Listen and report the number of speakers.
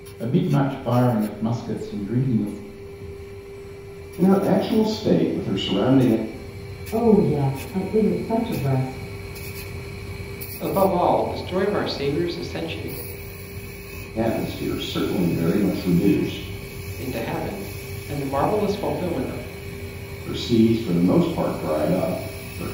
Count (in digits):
4